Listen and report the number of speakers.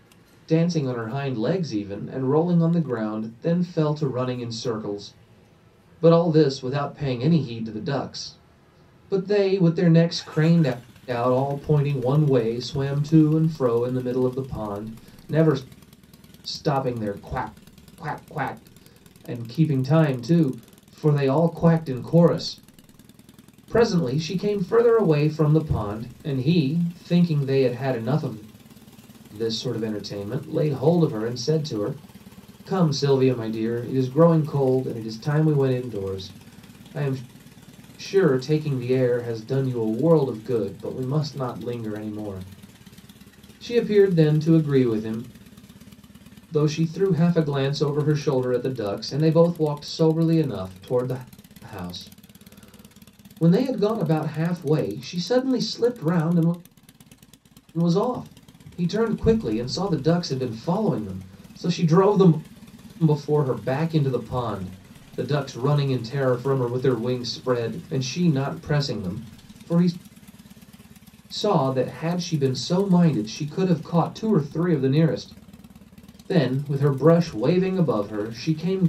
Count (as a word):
one